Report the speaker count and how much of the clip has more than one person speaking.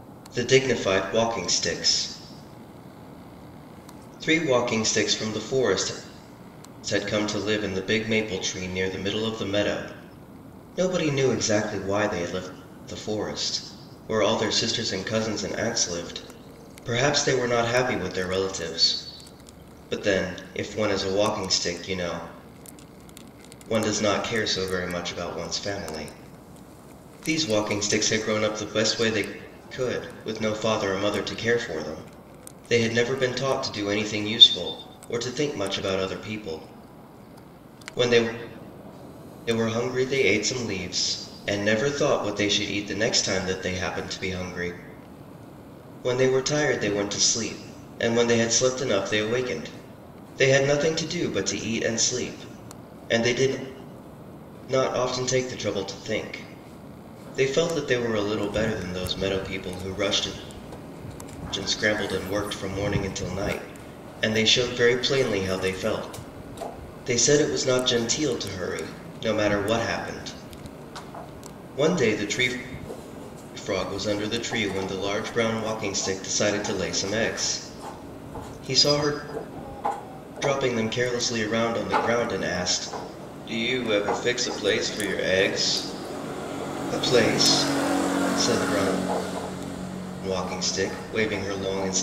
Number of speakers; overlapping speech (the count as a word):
one, no overlap